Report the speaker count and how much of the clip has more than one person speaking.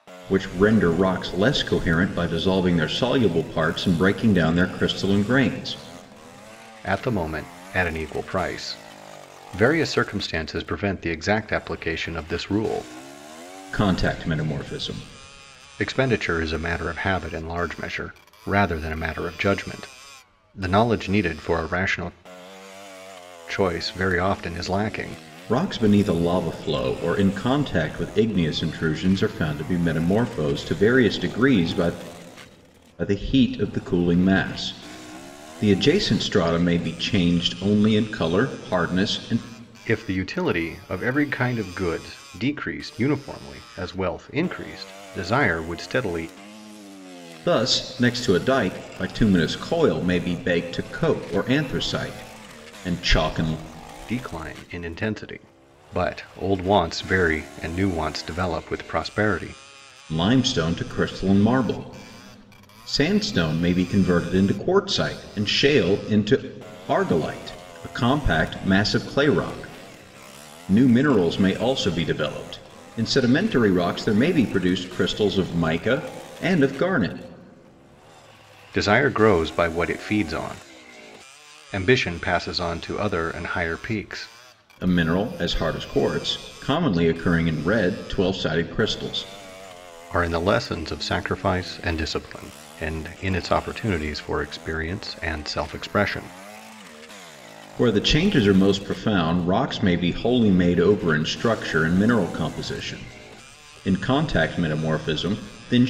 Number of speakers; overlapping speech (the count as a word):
two, no overlap